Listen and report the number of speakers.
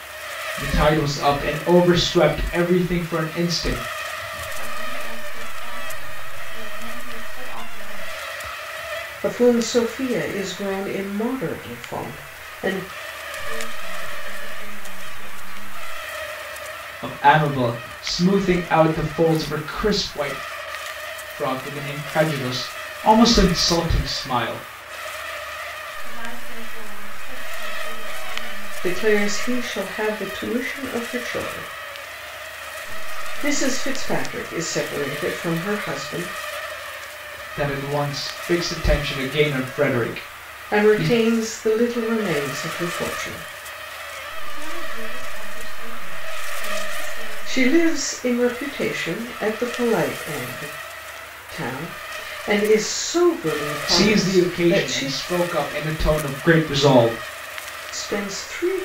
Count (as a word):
three